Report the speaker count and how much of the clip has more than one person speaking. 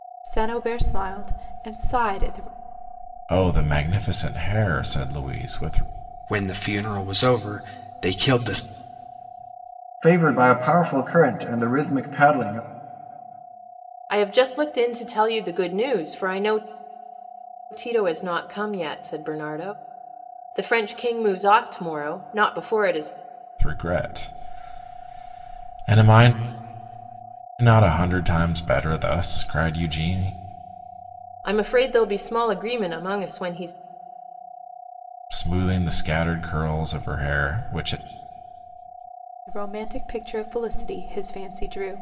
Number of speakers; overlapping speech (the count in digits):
5, no overlap